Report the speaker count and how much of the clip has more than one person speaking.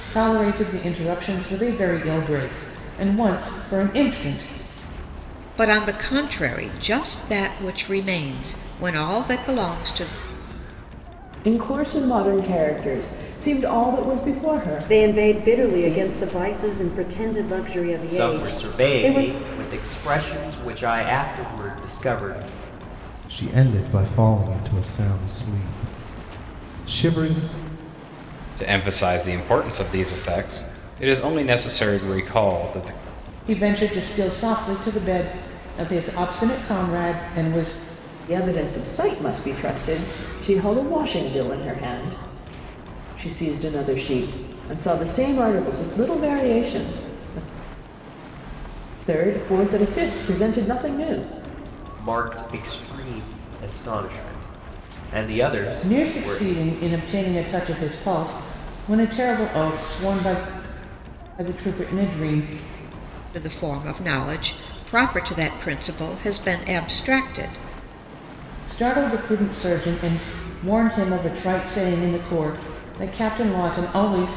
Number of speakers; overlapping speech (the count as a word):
seven, about 4%